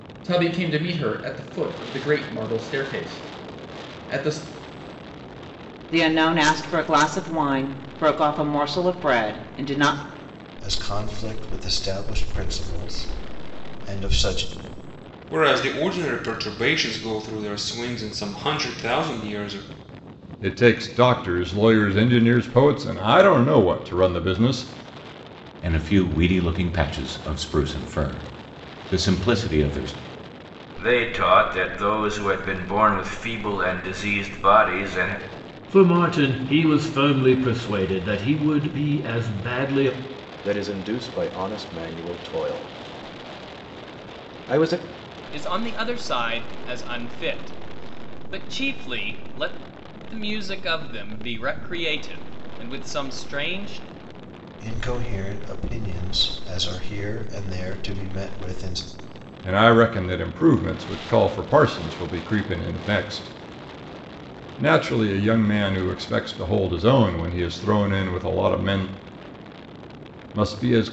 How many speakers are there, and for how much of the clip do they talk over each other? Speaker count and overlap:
10, no overlap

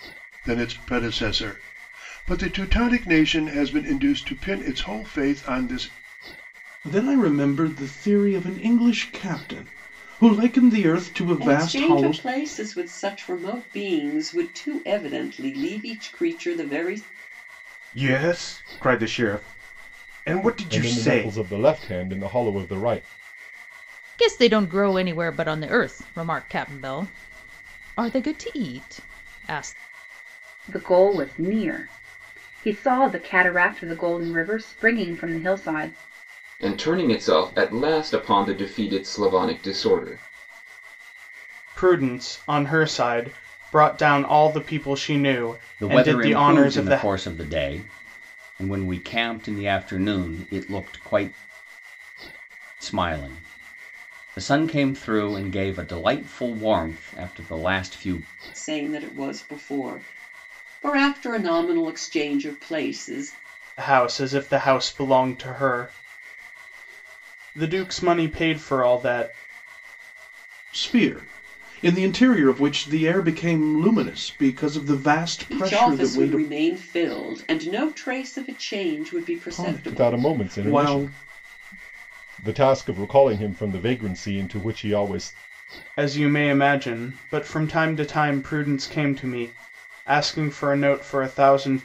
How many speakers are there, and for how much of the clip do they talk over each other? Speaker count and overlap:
10, about 6%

